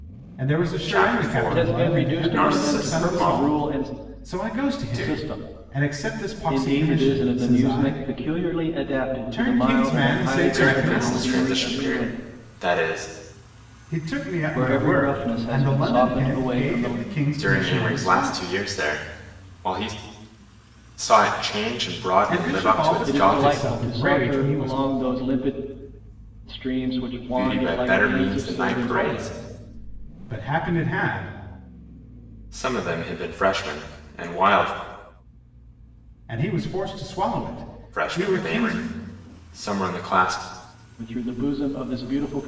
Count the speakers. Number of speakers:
3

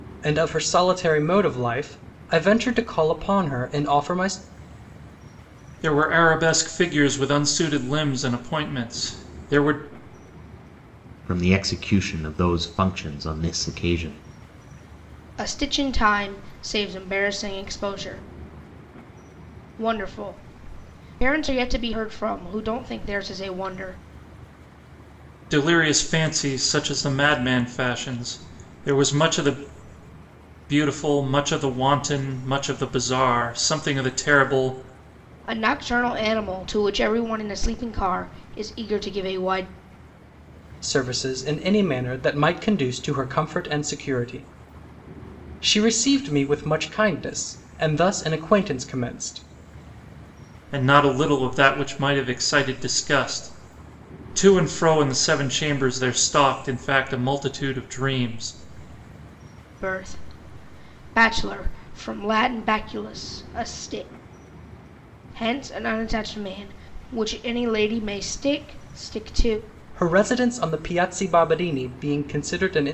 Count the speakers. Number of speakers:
4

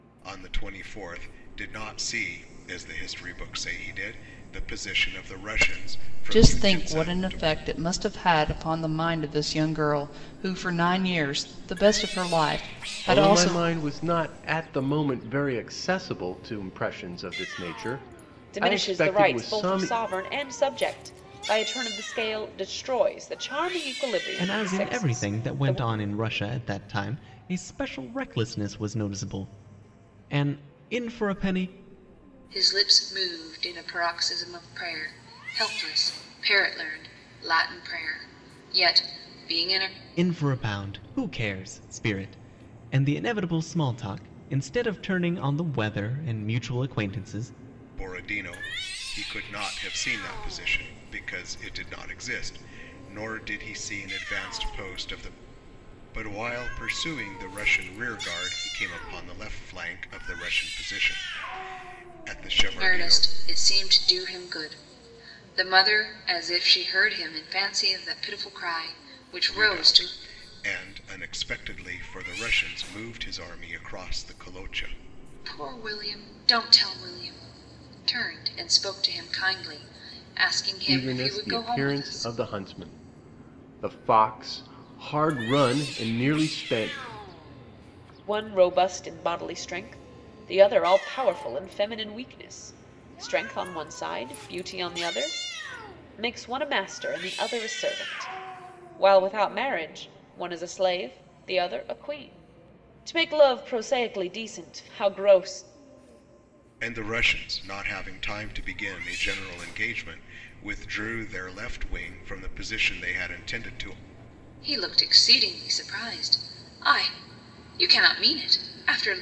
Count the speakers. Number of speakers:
6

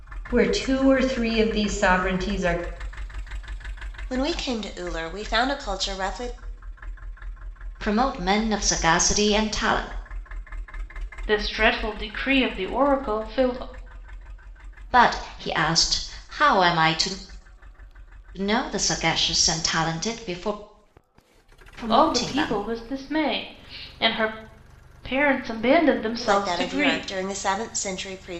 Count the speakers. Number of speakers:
4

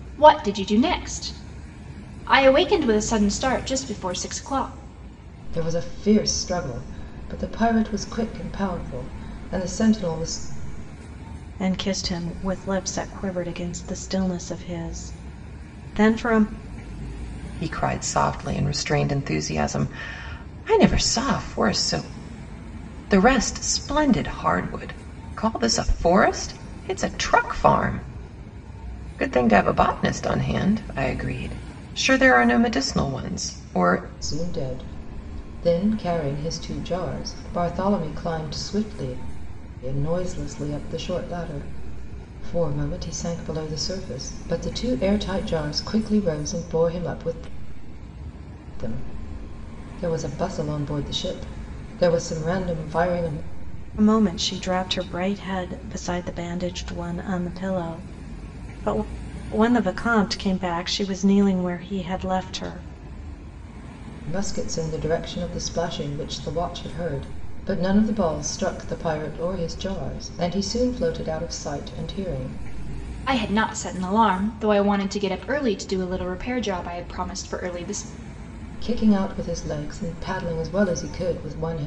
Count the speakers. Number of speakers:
4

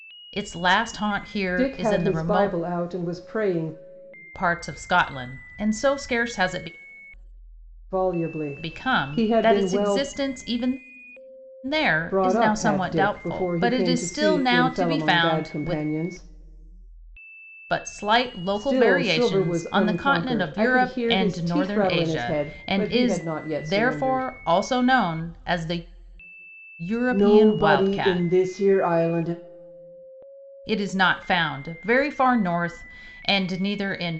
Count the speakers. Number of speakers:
2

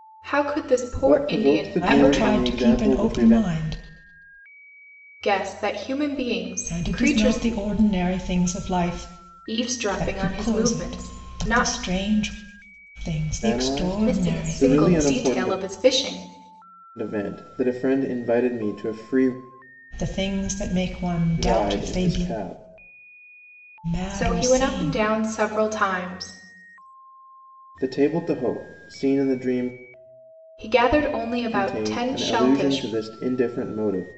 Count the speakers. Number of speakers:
3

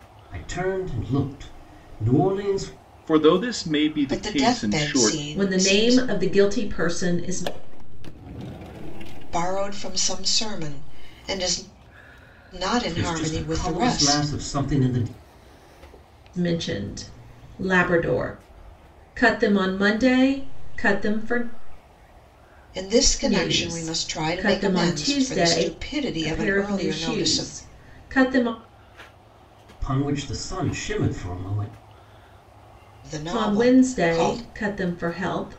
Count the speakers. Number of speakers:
5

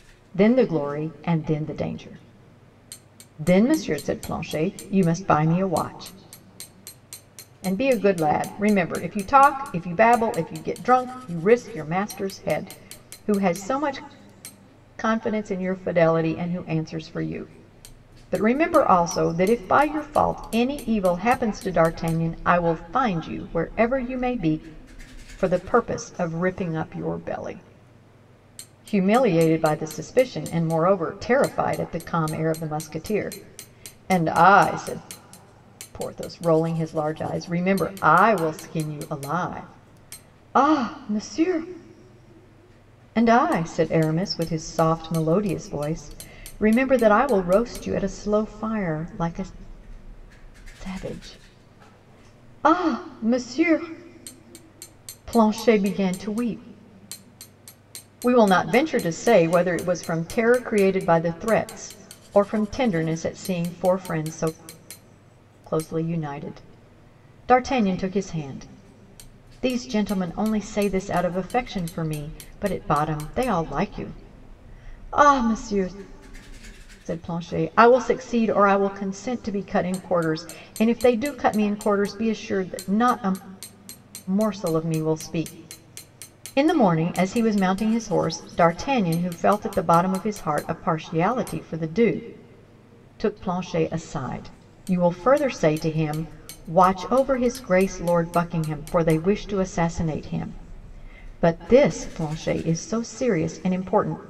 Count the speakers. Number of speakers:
1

